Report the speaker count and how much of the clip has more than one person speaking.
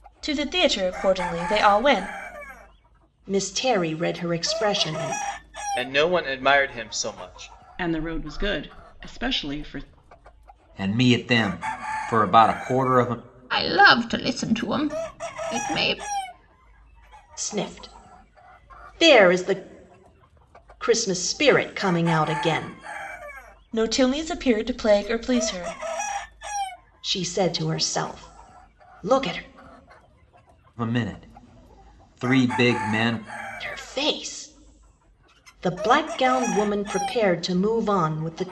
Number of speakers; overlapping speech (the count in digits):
6, no overlap